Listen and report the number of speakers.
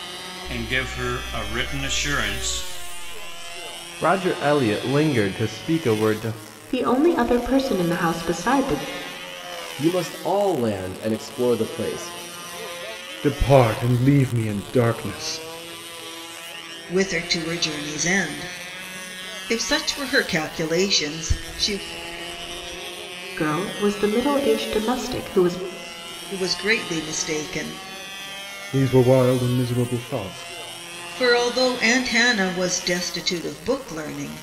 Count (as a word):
six